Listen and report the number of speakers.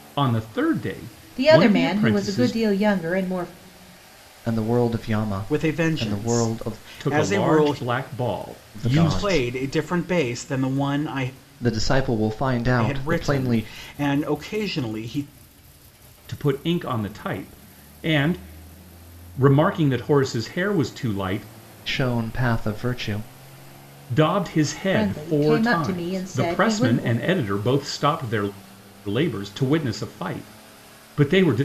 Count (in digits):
4